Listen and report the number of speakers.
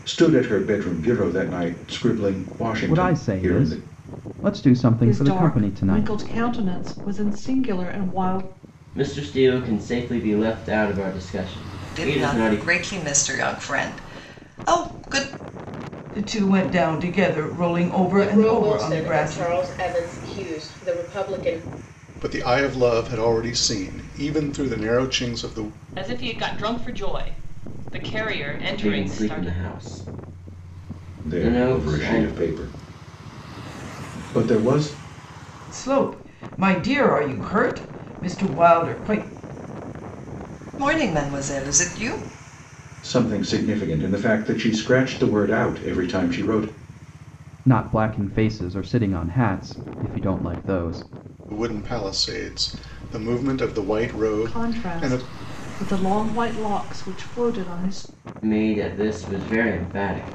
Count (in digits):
9